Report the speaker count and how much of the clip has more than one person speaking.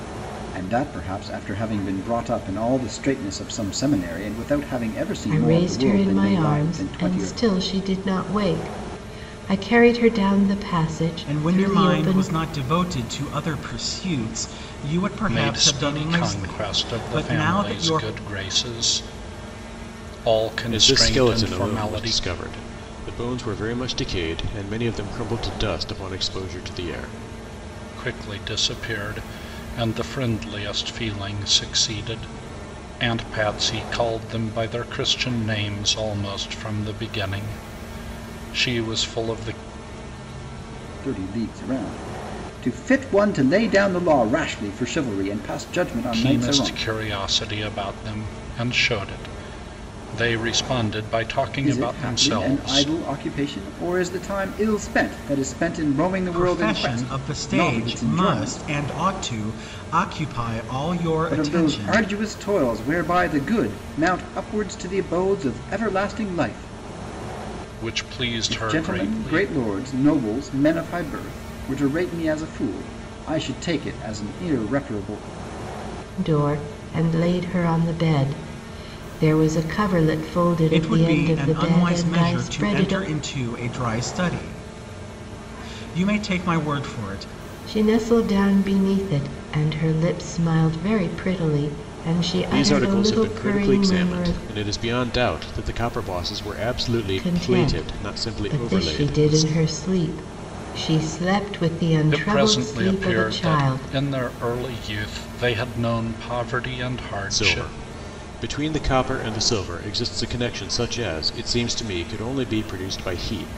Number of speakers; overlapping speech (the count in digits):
5, about 20%